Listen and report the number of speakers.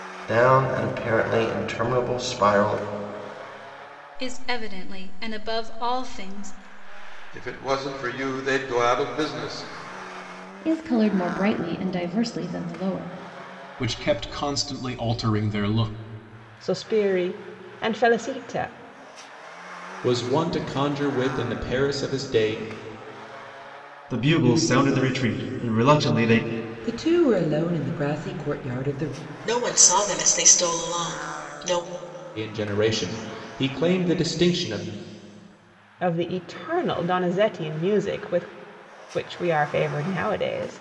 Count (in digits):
10